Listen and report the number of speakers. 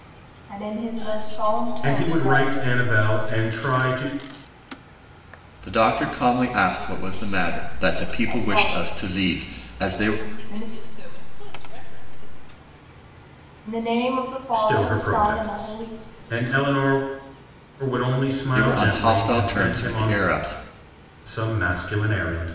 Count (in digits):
4